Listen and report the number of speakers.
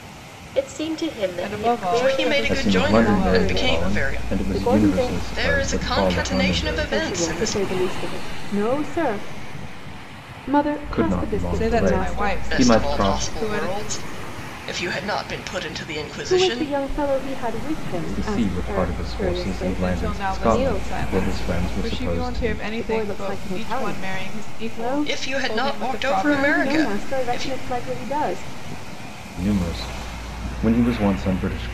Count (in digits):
5